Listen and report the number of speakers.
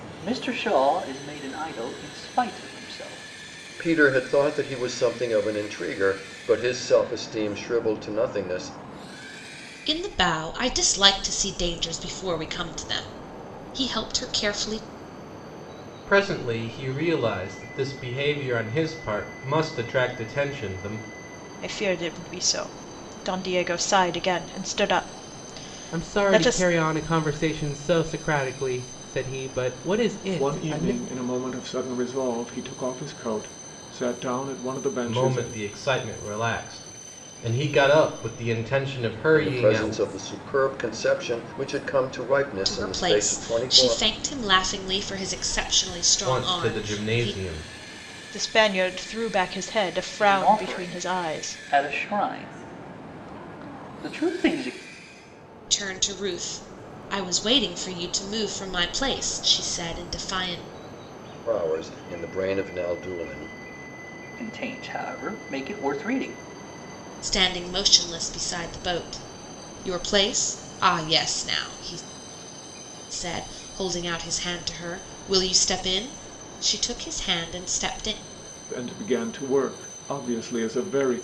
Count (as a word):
seven